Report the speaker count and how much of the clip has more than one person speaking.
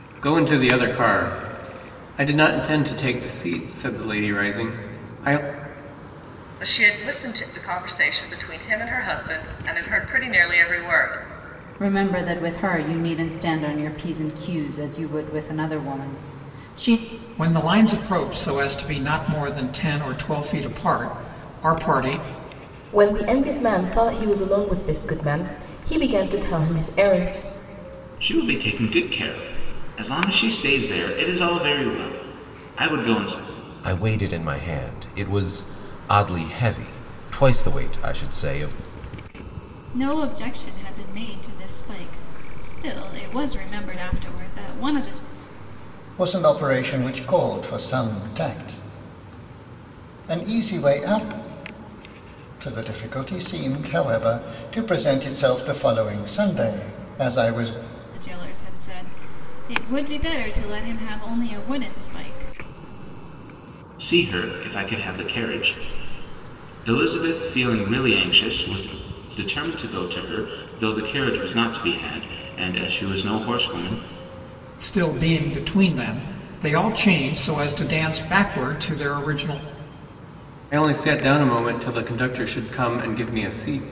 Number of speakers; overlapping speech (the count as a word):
nine, no overlap